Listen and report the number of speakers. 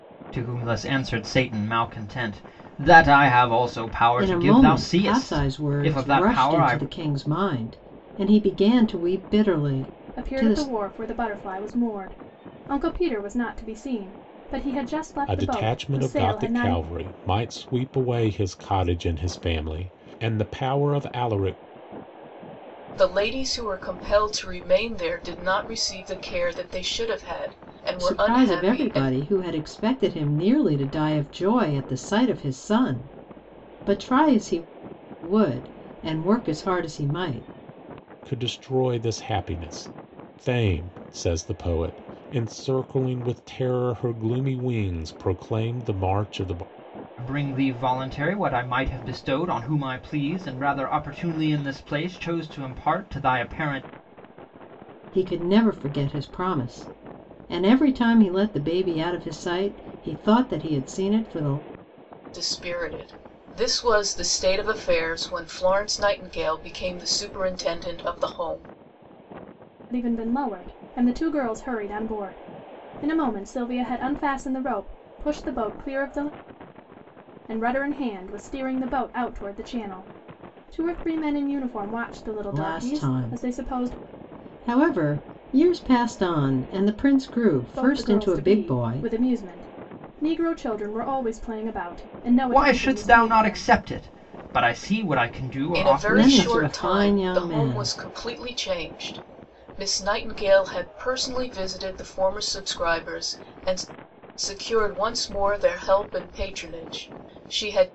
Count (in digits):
5